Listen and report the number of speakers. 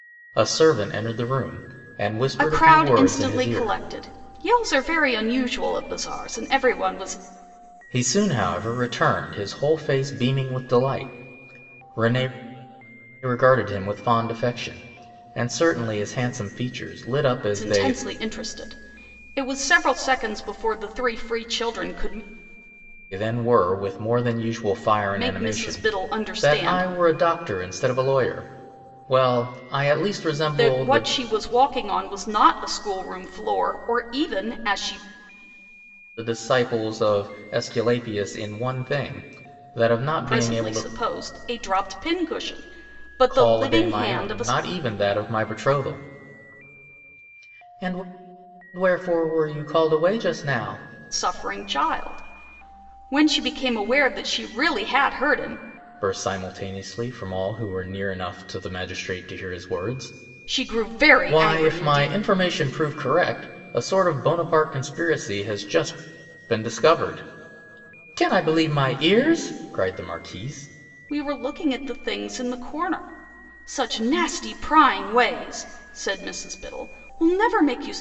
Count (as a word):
two